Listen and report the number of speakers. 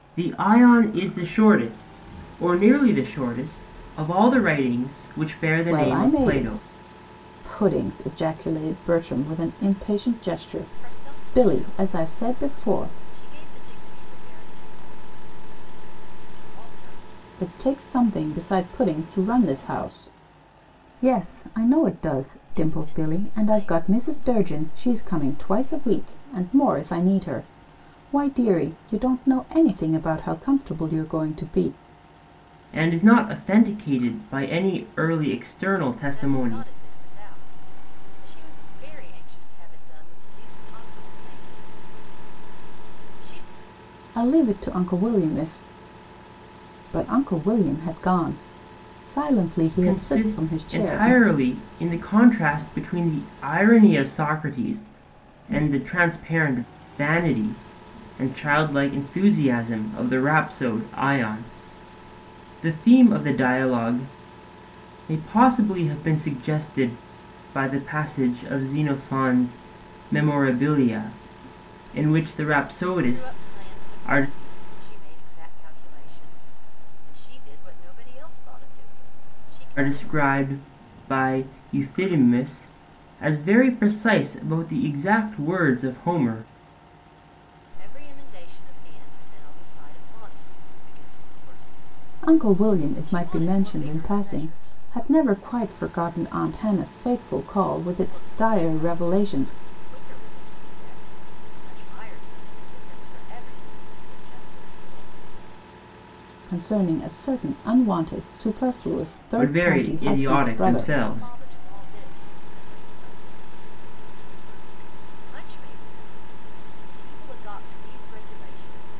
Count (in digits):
3